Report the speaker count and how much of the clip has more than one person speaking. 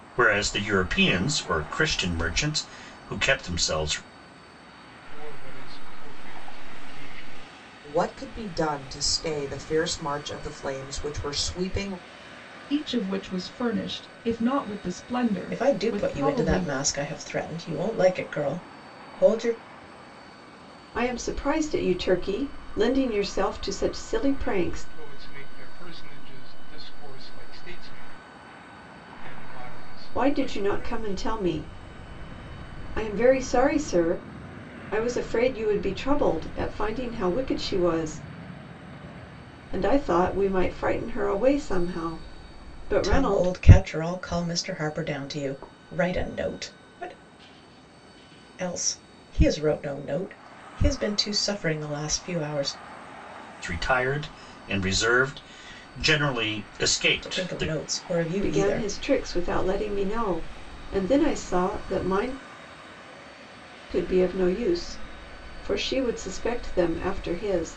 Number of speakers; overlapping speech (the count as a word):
six, about 7%